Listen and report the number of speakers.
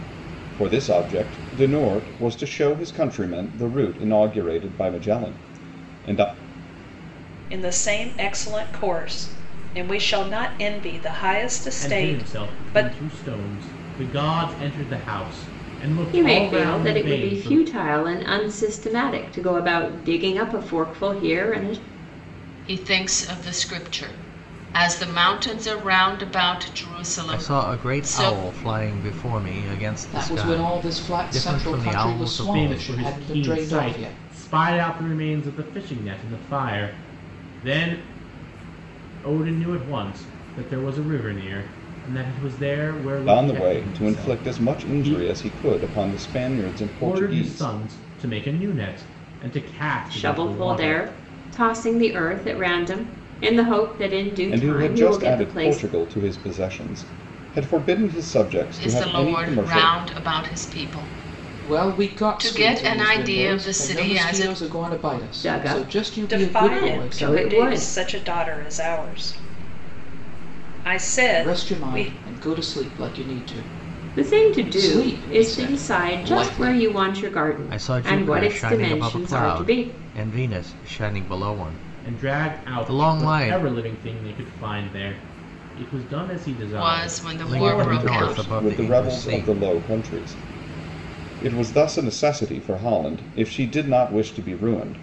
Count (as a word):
seven